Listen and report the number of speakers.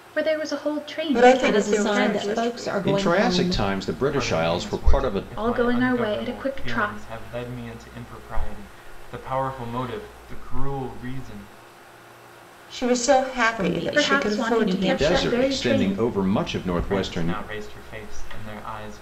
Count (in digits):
5